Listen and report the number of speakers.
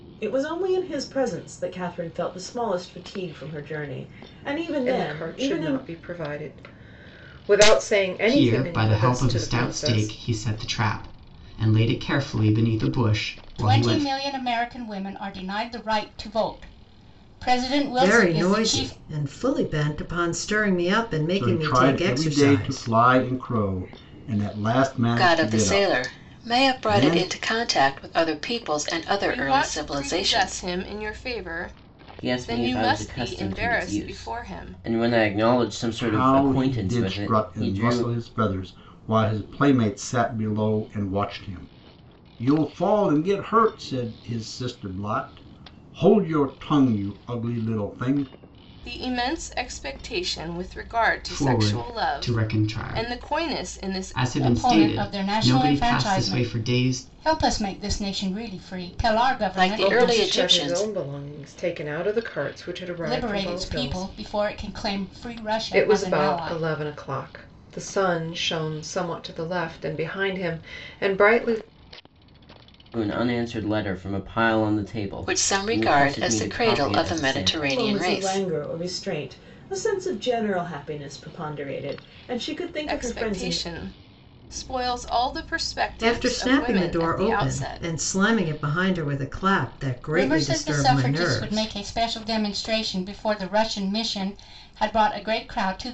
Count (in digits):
9